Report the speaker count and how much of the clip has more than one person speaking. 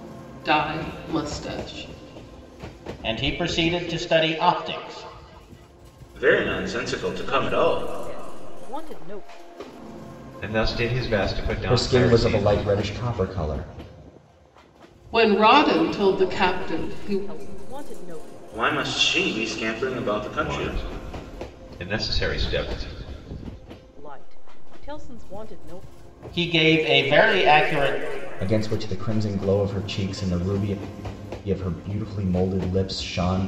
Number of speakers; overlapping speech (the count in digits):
6, about 15%